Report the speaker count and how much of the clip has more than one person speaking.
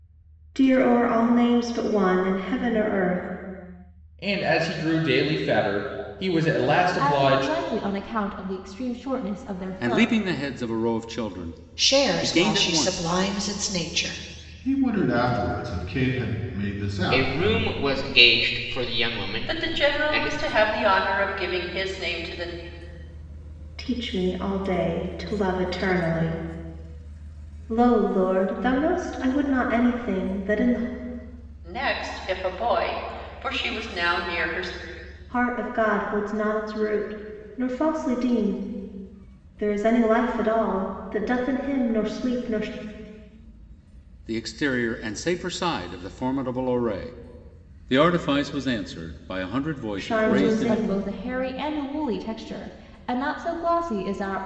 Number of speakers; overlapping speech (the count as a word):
eight, about 9%